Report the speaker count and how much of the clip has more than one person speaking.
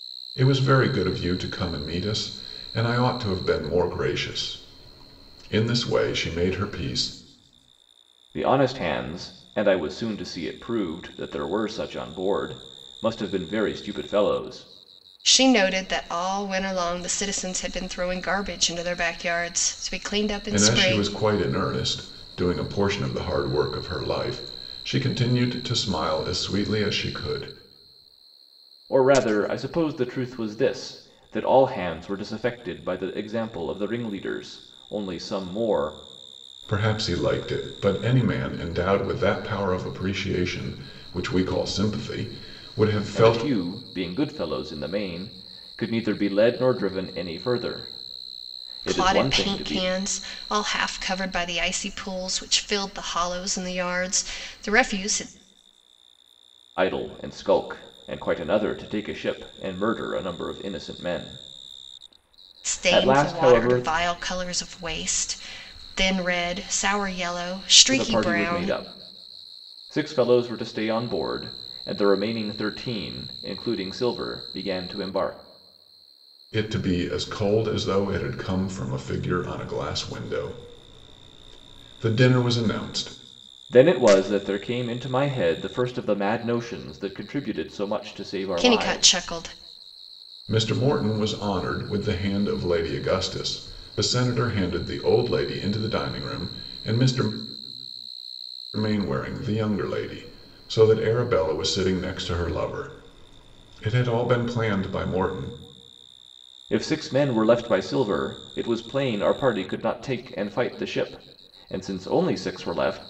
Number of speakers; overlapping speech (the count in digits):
3, about 4%